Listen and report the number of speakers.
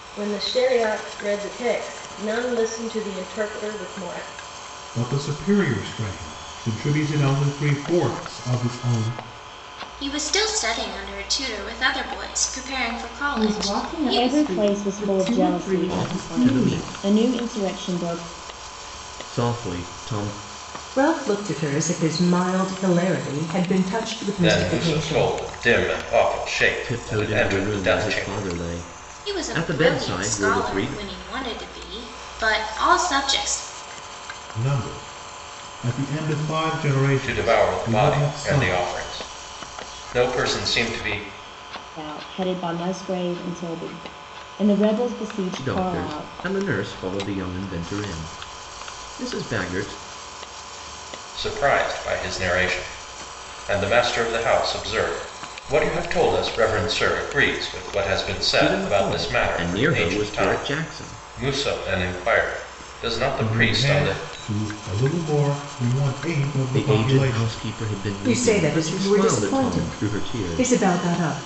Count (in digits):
8